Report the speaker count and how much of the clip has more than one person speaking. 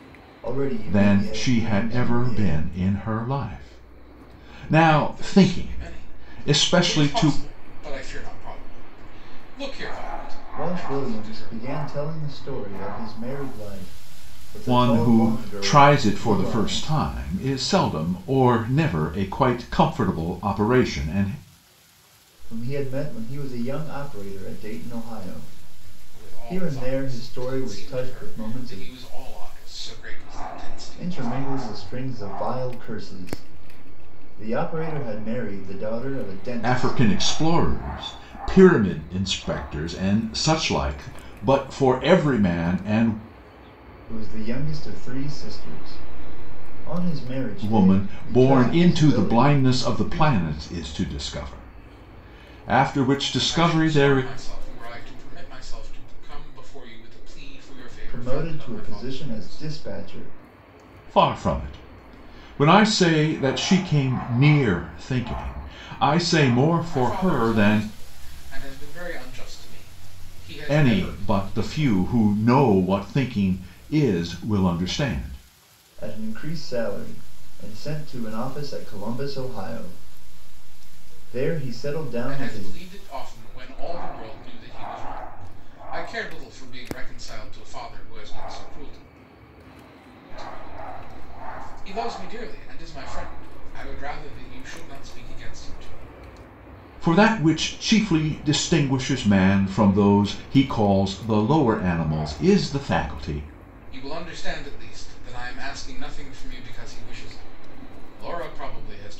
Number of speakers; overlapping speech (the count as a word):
three, about 19%